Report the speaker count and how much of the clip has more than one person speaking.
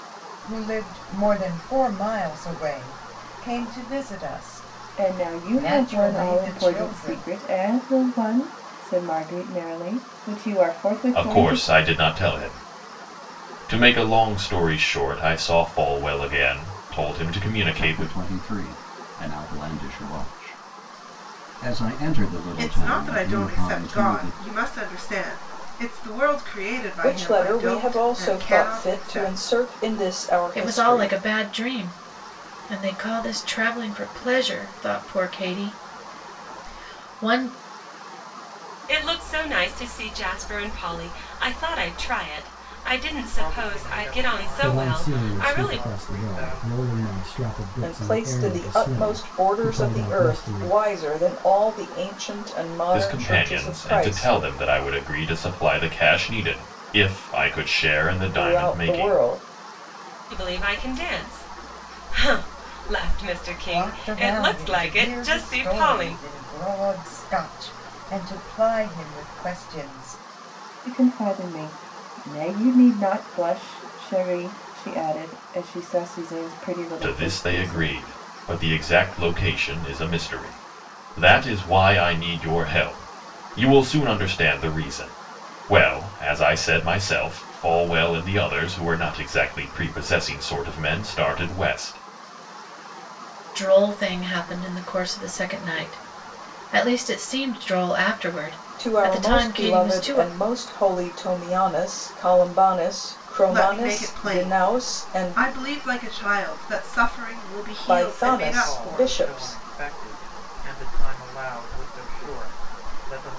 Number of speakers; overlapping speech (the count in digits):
10, about 24%